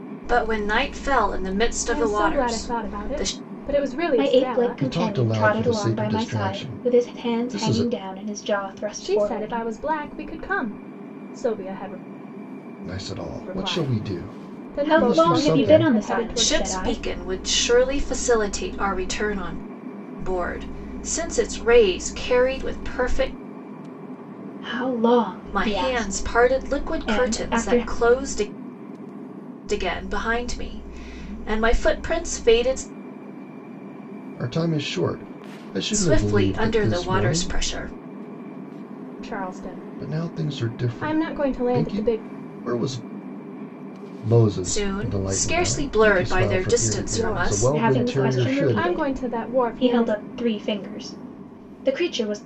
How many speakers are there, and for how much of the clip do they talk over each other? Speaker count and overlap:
4, about 41%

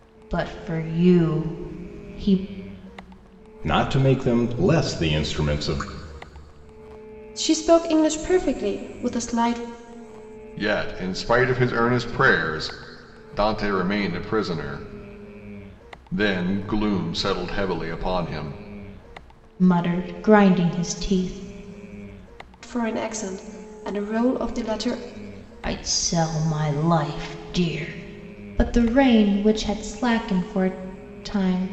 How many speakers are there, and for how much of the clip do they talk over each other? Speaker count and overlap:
4, no overlap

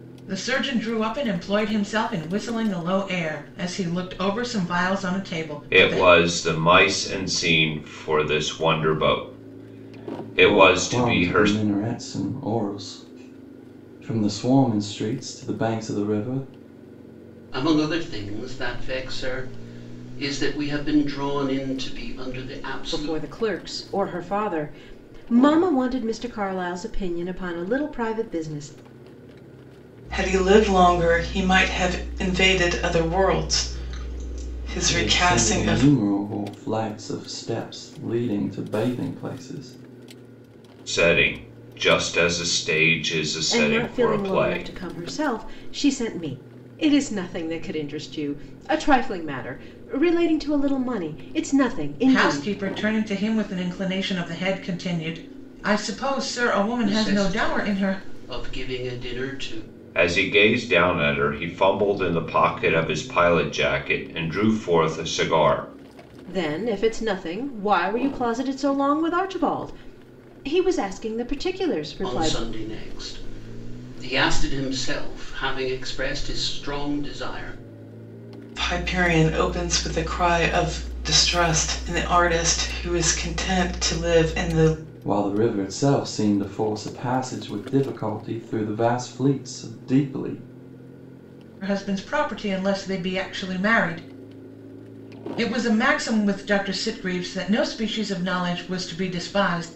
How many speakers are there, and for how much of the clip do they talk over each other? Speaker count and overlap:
6, about 6%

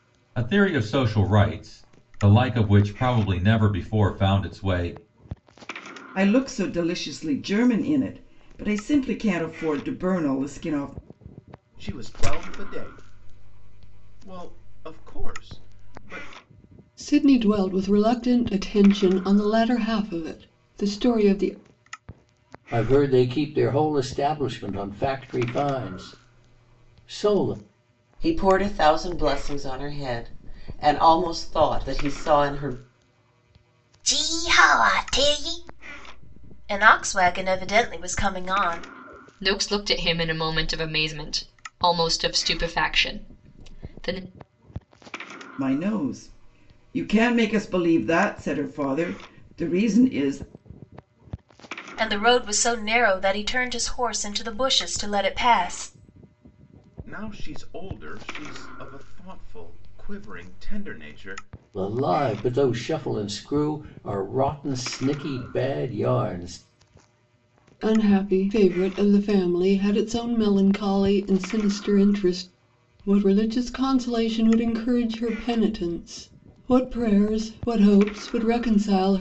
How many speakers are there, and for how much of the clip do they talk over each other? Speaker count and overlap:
8, no overlap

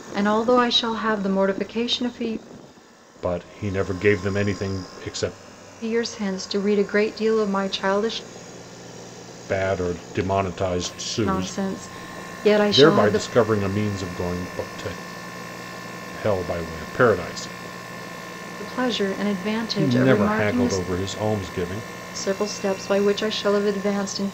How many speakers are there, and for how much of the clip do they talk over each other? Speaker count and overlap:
2, about 9%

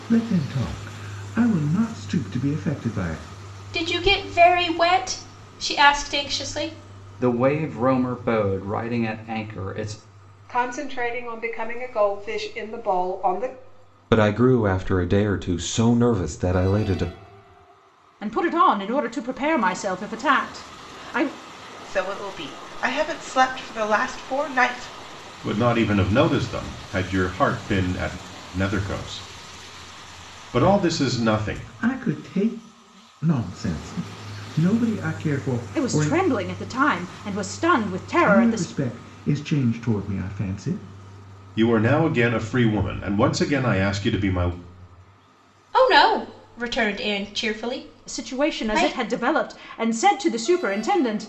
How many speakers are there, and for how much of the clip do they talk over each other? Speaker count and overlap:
8, about 6%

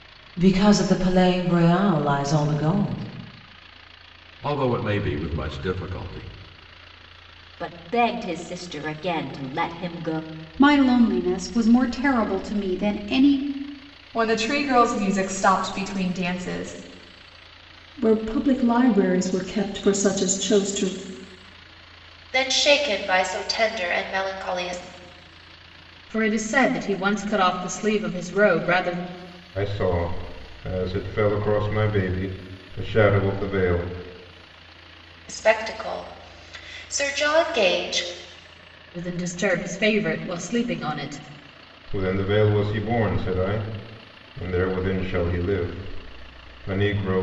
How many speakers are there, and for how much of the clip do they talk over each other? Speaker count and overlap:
9, no overlap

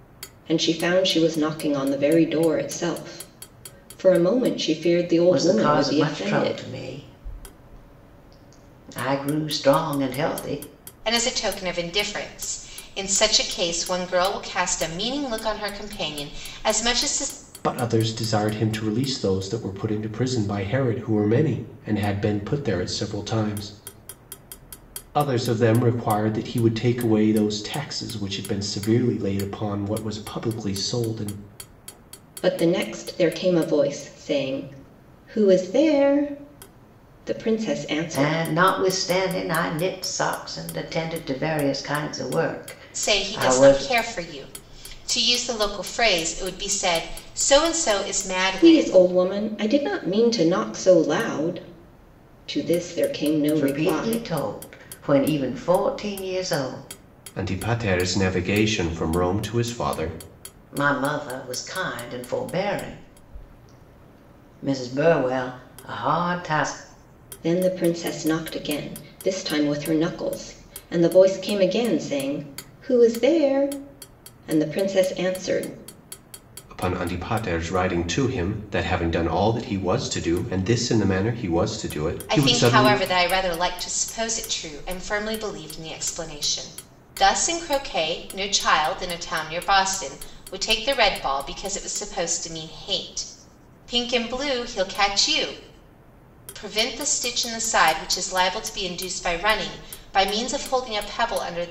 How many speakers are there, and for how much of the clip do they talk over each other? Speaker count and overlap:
4, about 5%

